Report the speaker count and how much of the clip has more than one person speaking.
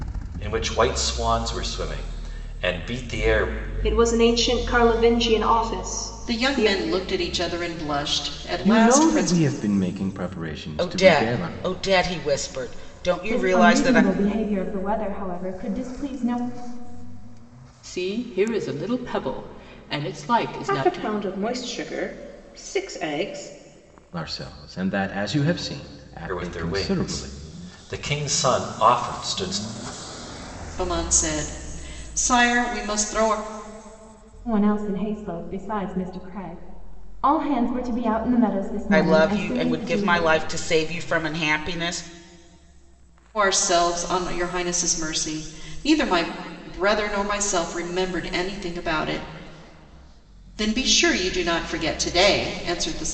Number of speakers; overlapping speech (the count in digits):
8, about 11%